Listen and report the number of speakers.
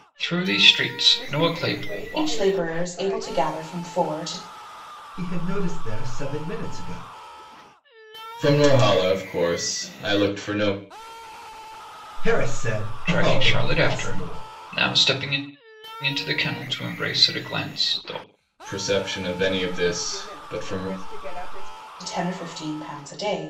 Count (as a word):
five